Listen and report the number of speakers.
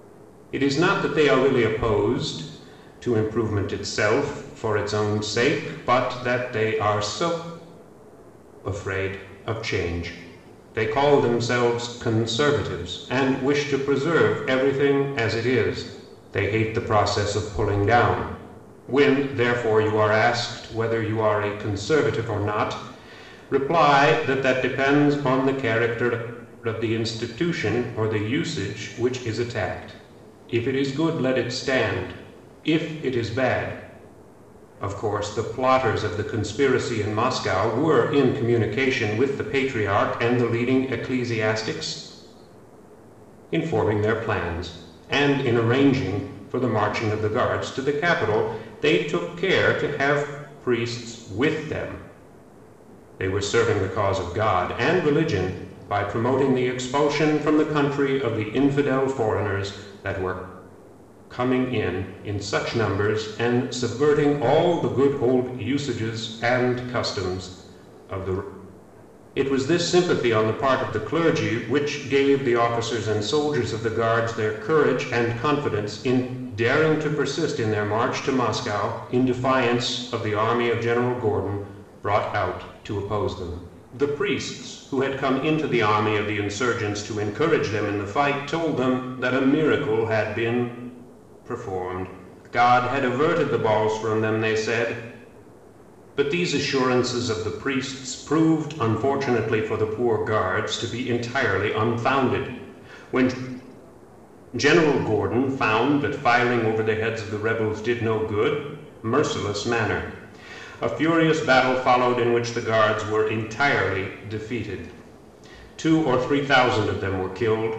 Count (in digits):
1